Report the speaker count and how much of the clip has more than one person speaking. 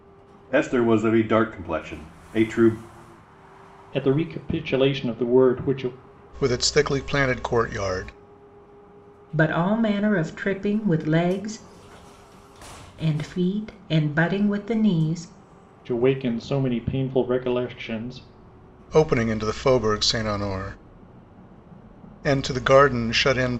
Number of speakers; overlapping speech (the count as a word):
four, no overlap